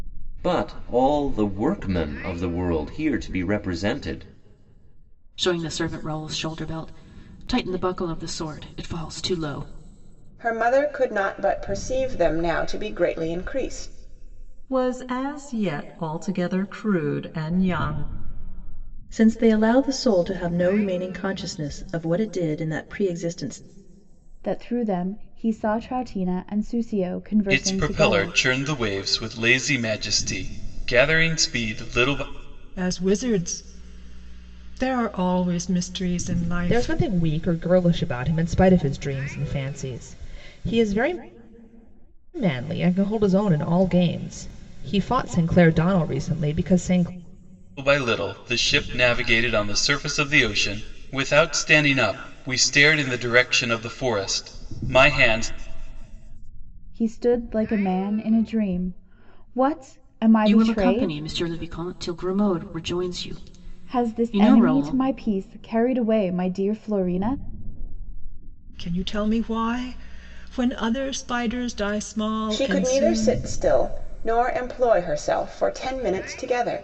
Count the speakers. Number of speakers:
9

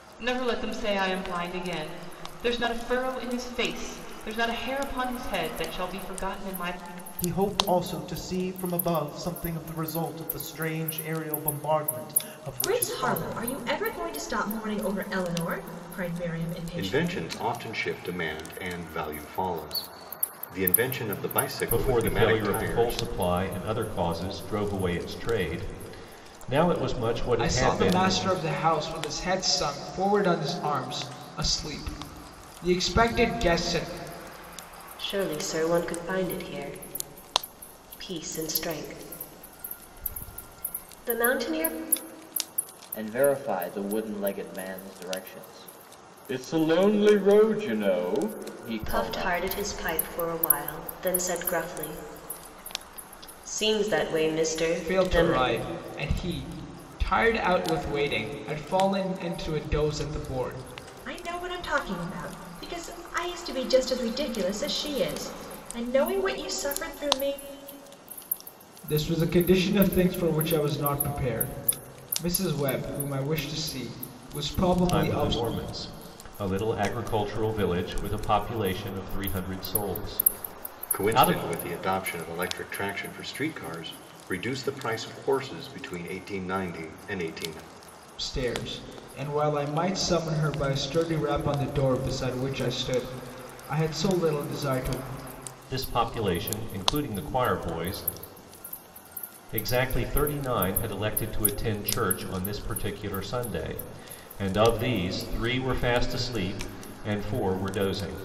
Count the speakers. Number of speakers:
8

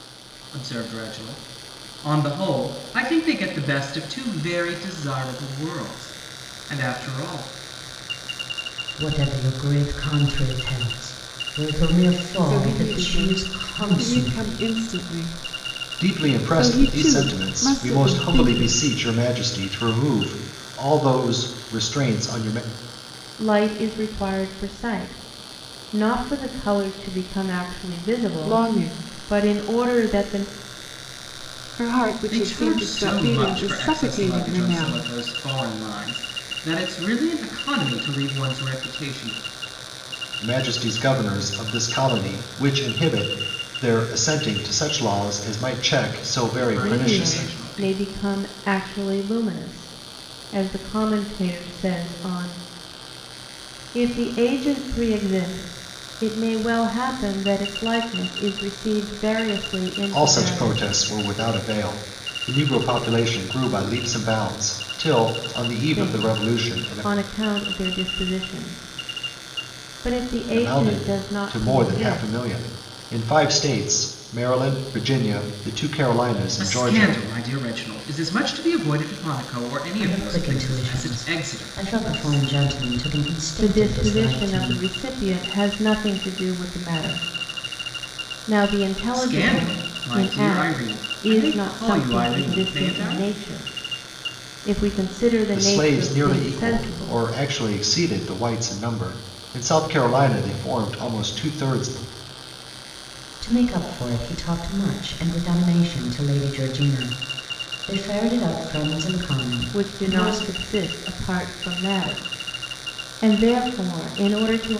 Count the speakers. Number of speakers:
5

